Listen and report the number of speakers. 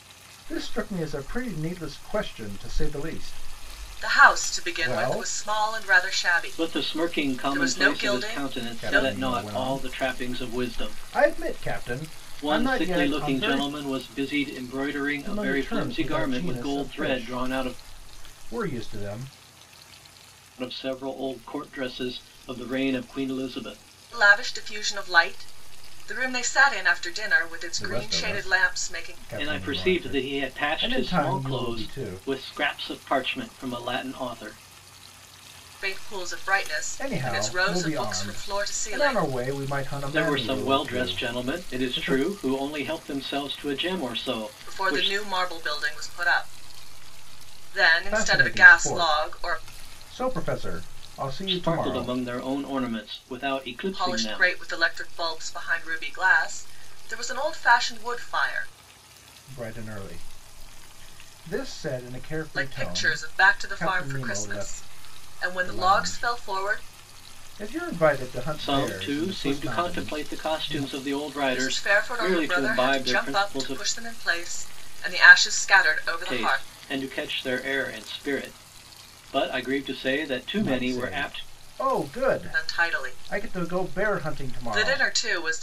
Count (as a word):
three